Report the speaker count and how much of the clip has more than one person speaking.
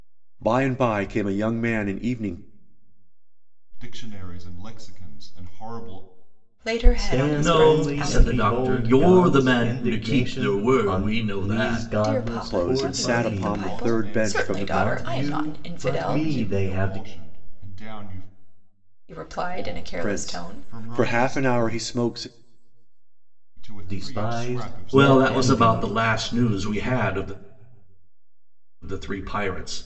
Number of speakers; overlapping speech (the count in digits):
5, about 48%